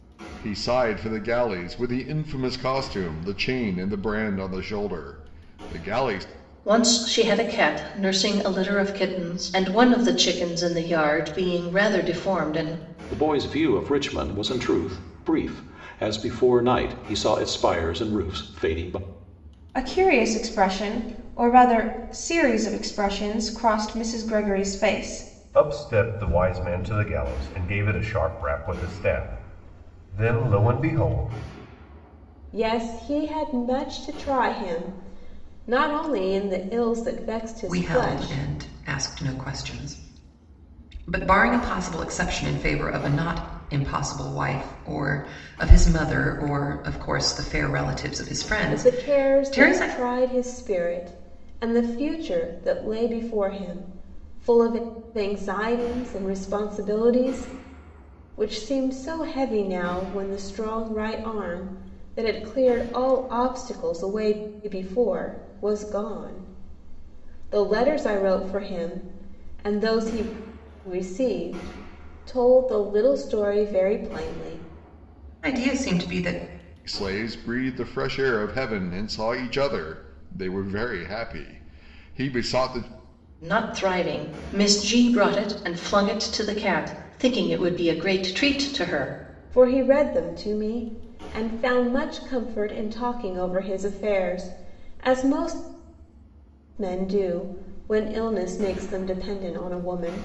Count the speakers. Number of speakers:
seven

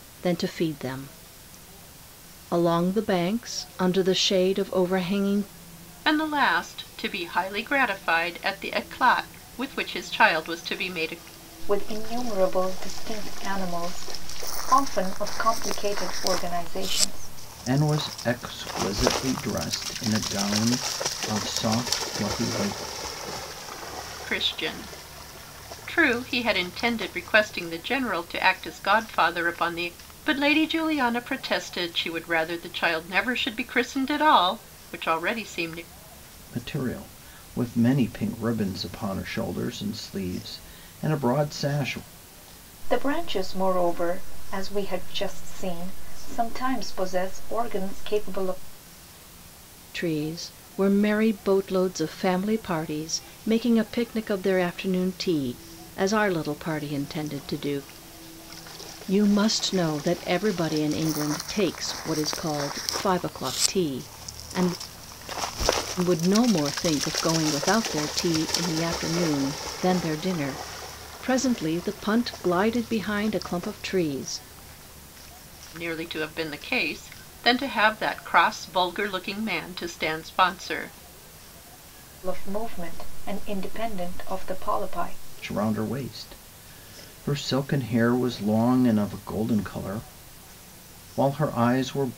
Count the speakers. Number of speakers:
four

